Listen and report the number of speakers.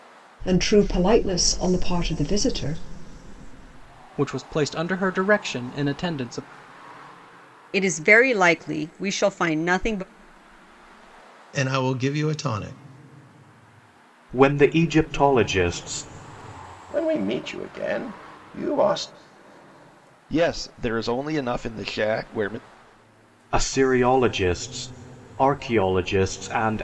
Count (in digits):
7